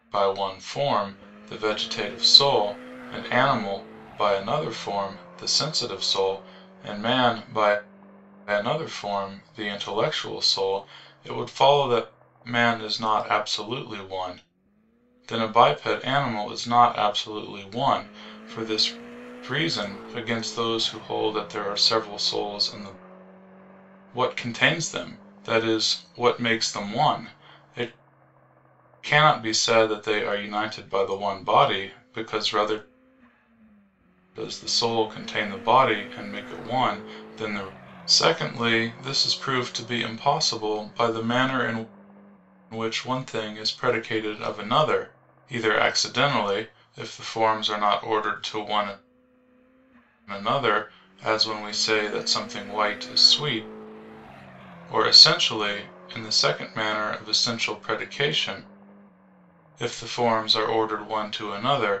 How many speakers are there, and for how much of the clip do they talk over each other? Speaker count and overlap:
1, no overlap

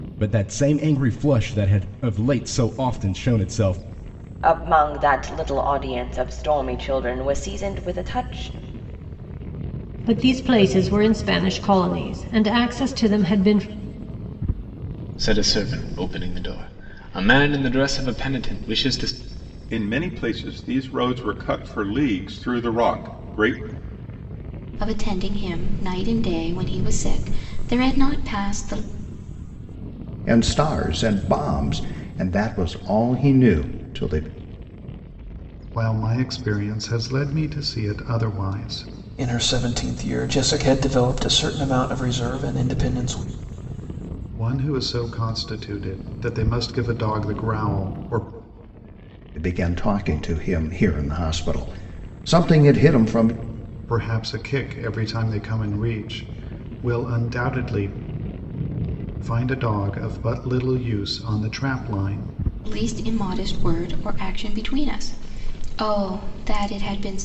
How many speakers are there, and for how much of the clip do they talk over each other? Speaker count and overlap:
9, no overlap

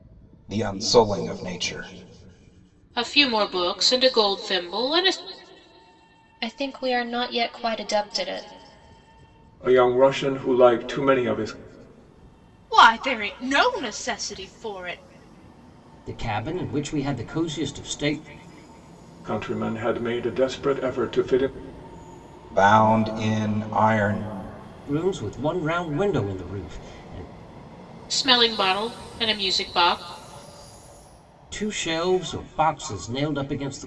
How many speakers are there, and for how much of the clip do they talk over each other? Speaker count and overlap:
6, no overlap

